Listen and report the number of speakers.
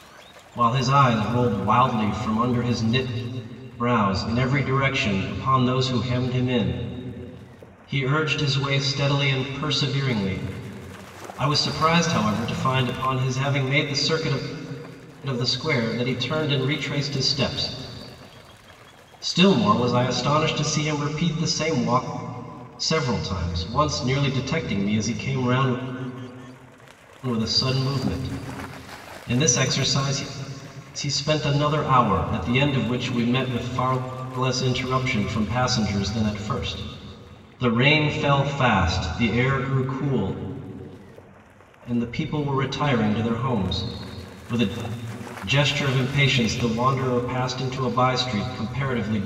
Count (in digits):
1